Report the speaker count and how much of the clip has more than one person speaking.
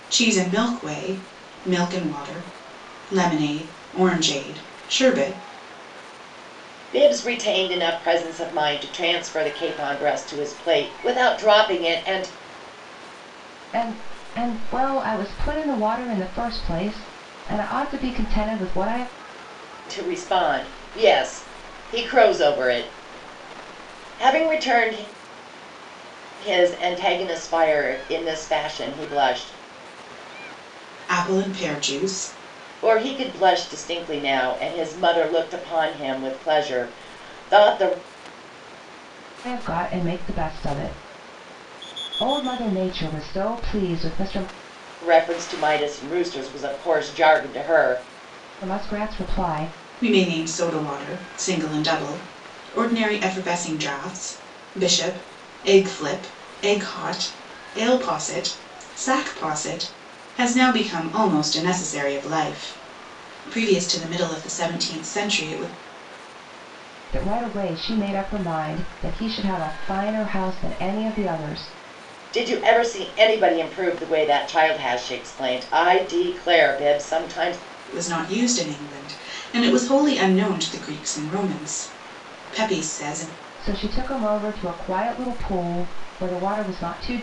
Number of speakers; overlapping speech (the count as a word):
three, no overlap